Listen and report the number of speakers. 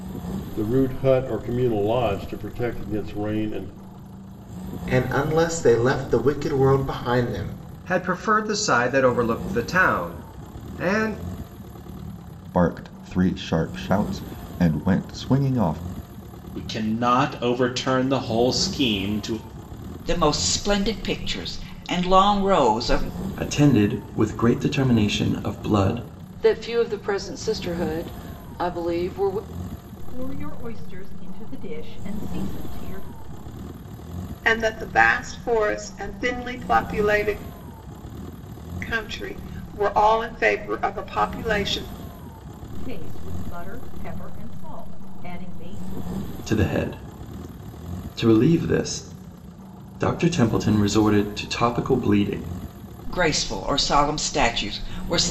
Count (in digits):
10